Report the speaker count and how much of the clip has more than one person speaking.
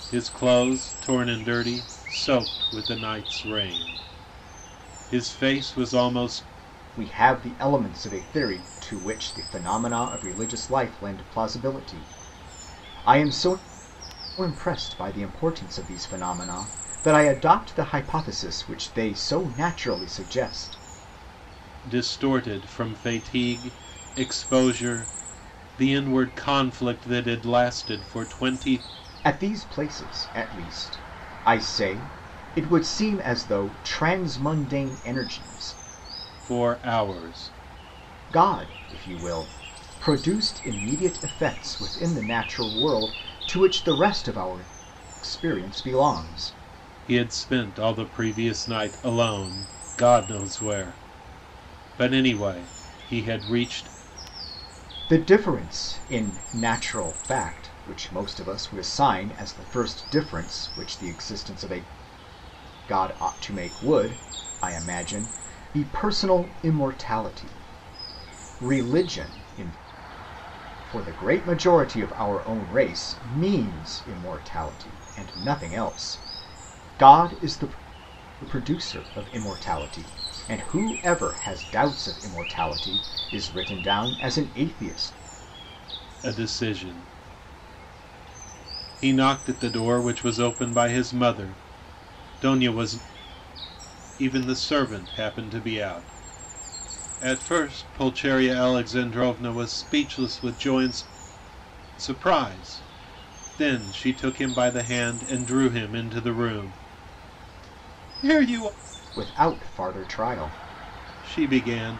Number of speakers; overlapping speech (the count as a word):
two, no overlap